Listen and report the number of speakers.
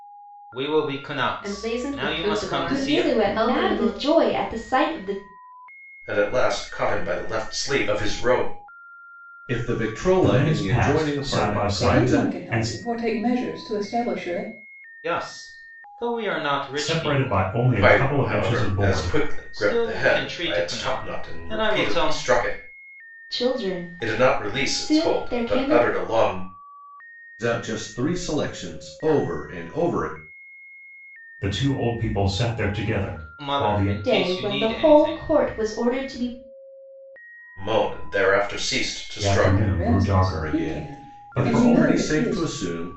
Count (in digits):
7